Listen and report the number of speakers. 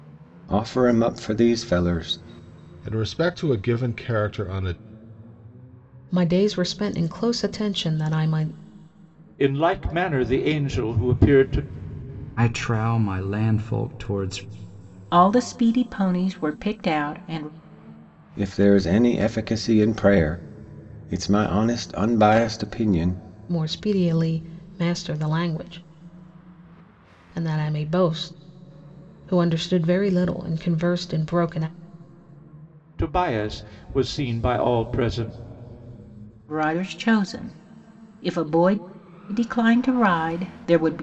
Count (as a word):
six